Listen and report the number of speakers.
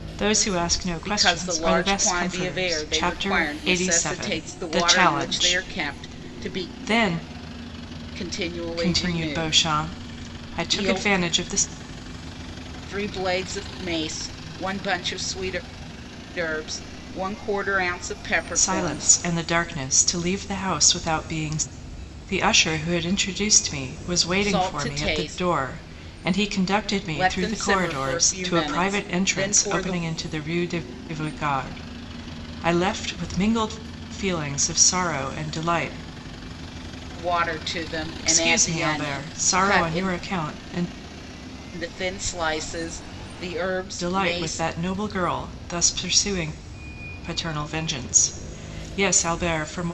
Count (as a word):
two